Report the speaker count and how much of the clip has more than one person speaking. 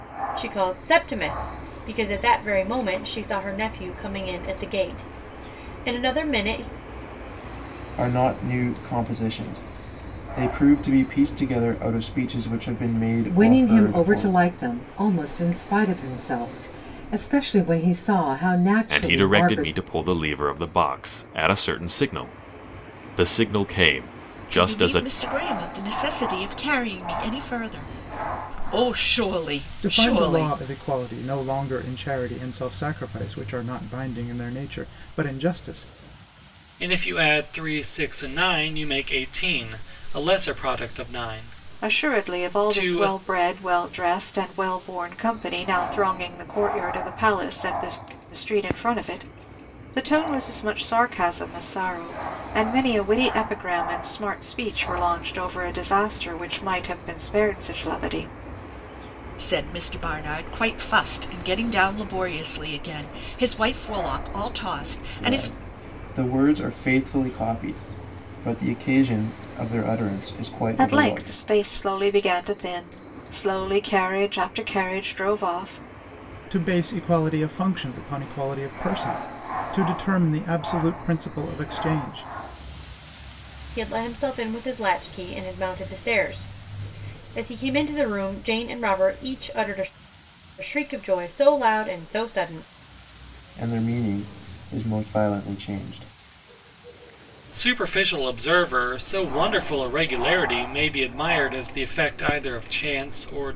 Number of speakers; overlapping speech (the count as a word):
eight, about 6%